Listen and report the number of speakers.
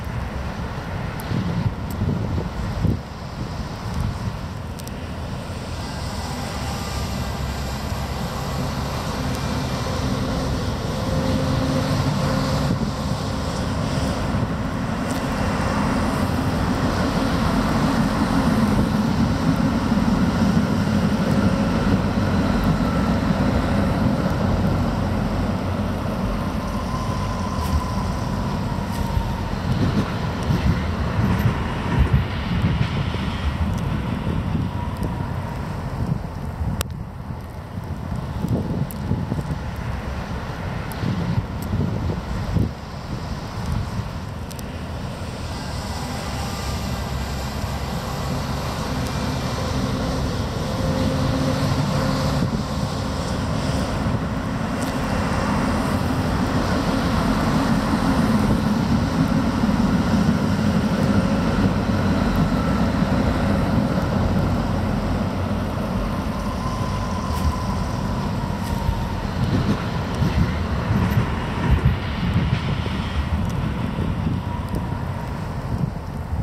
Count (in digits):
0